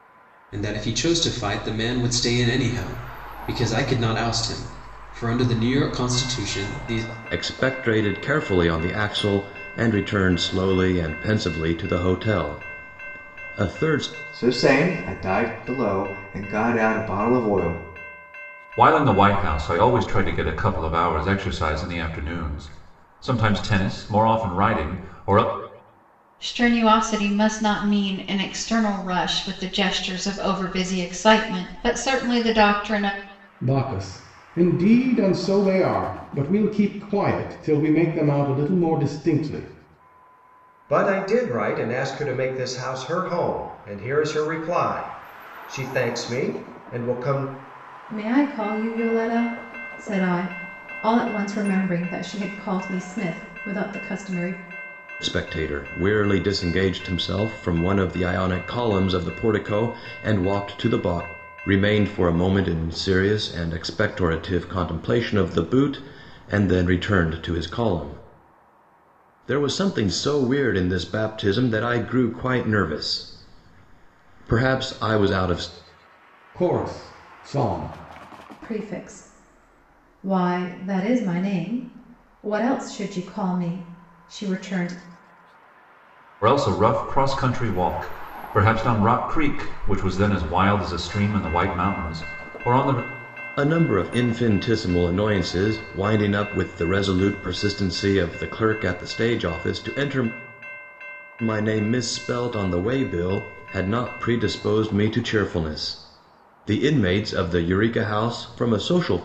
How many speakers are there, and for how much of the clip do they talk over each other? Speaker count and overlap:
8, no overlap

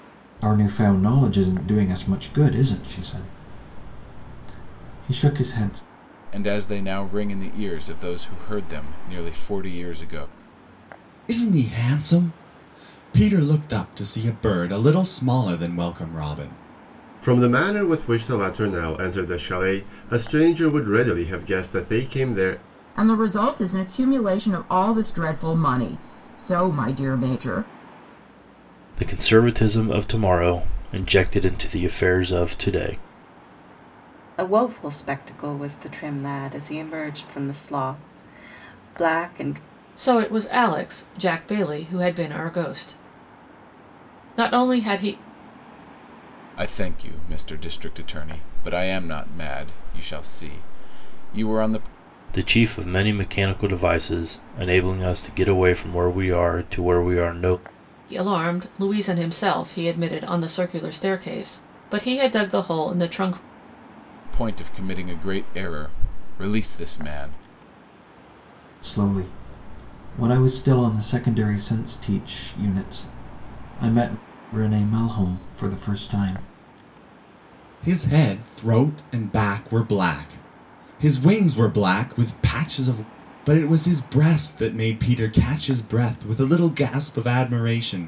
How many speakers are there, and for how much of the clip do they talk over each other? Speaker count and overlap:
8, no overlap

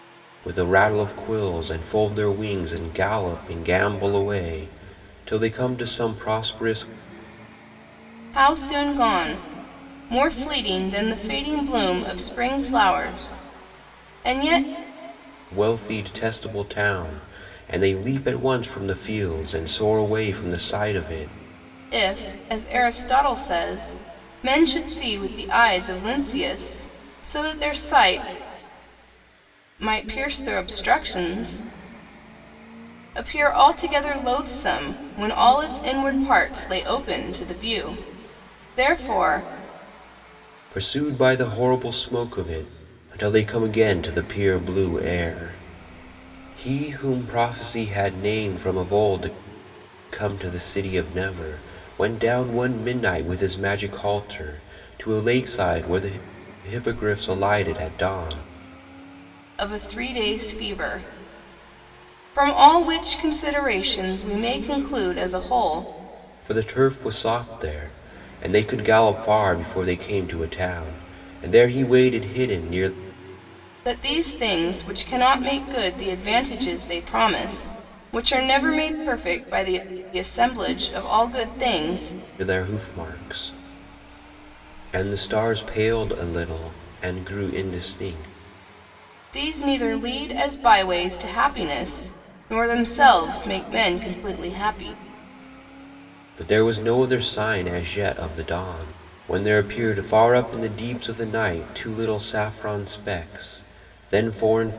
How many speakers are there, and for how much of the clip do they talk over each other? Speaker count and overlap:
2, no overlap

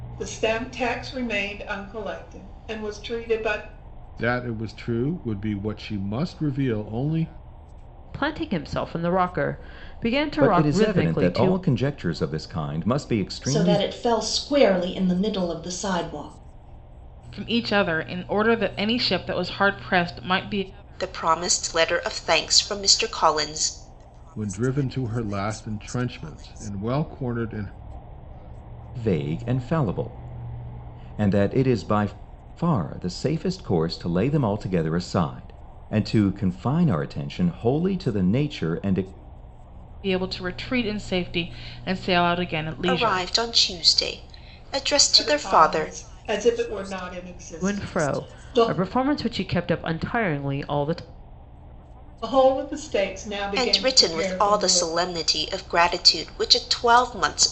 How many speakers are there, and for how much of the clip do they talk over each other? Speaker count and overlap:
7, about 9%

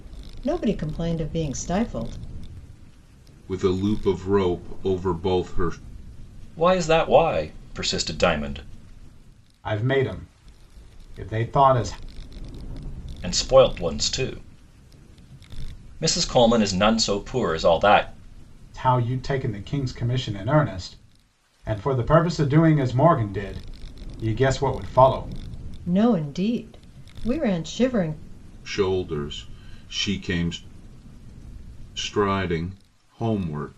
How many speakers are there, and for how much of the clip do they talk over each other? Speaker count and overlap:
4, no overlap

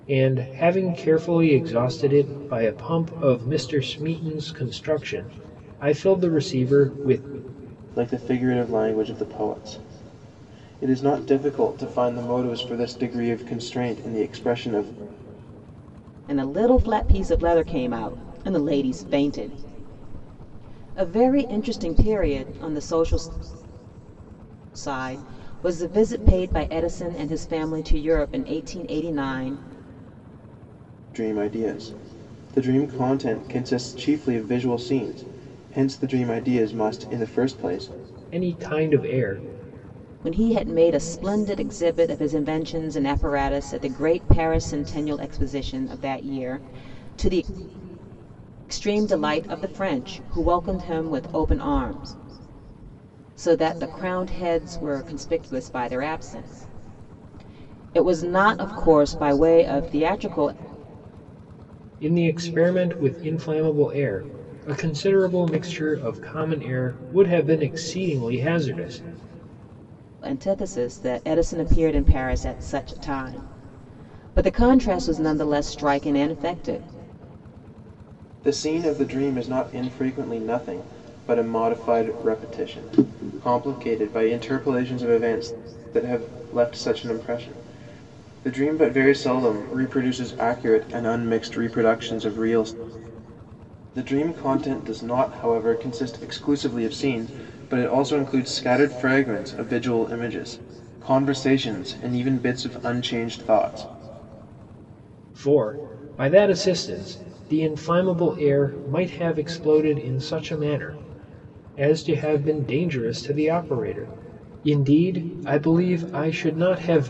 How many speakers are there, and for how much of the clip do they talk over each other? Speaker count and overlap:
3, no overlap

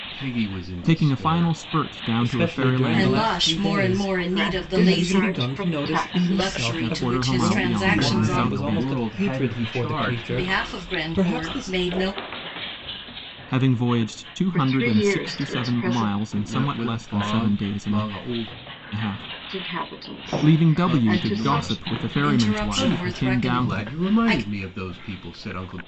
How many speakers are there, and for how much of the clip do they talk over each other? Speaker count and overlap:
5, about 73%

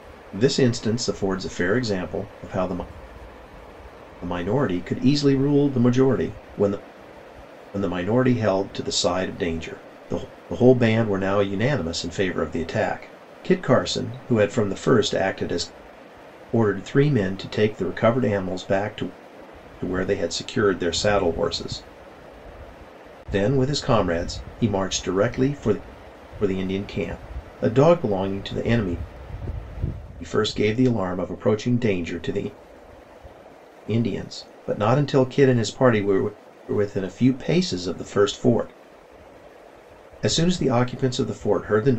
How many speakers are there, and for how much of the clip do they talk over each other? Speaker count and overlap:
1, no overlap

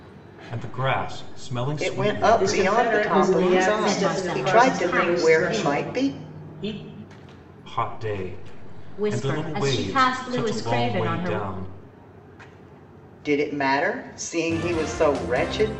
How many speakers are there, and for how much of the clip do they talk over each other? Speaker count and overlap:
4, about 42%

